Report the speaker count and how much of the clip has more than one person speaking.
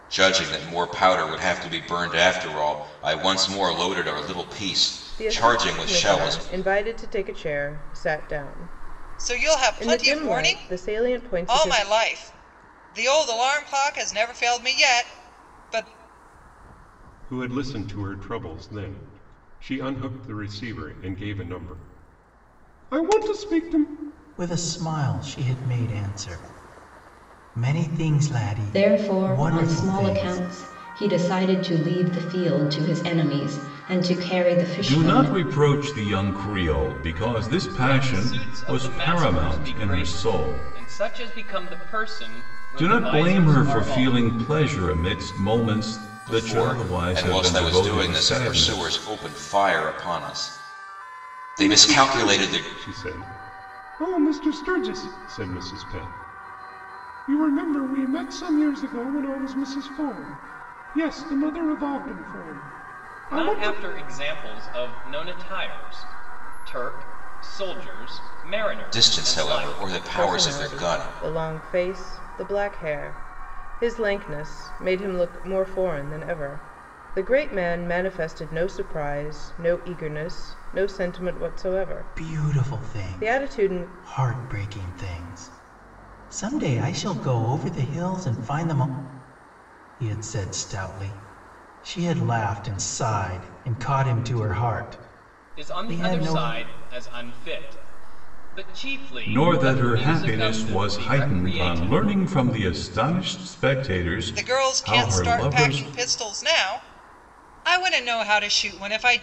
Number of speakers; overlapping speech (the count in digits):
8, about 22%